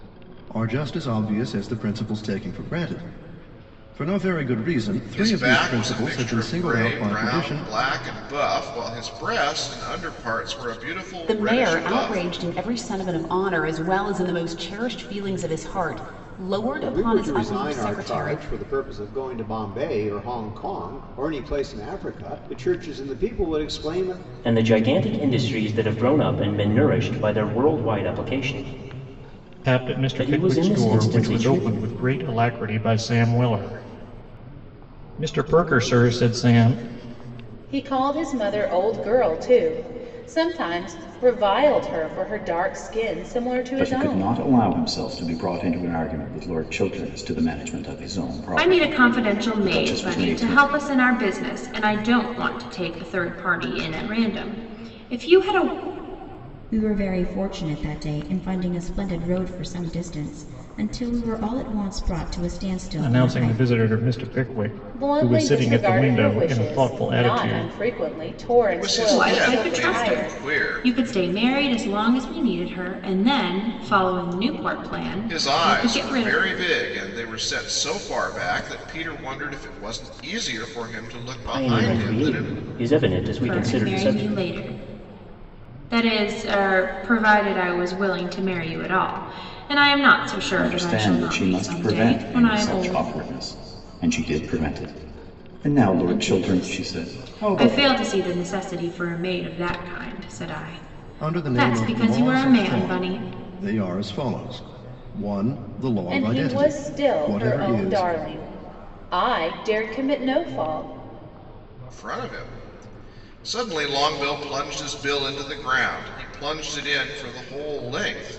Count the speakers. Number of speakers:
10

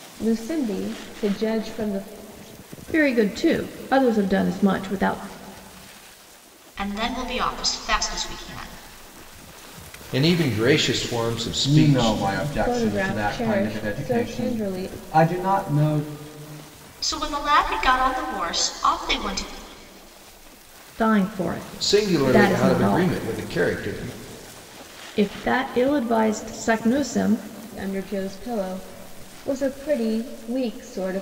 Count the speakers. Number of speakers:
5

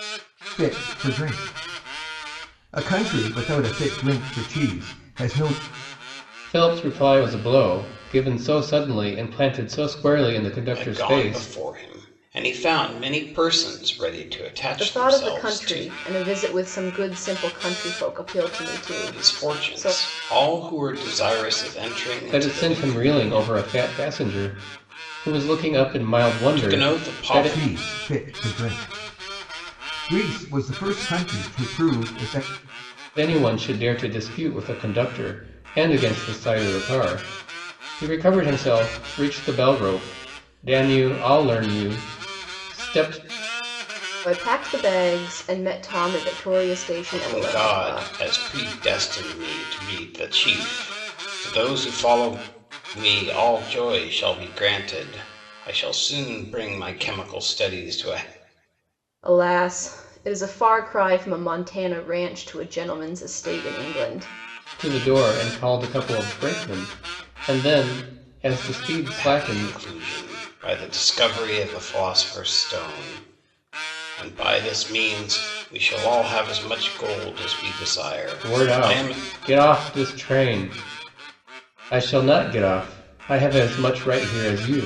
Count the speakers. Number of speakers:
4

